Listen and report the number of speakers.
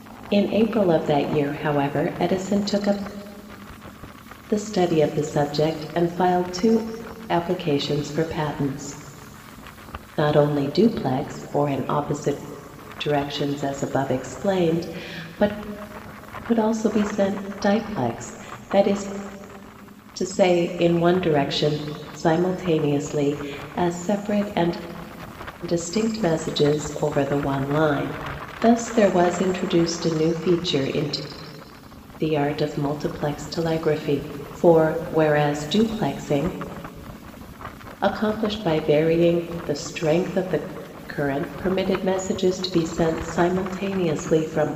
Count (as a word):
one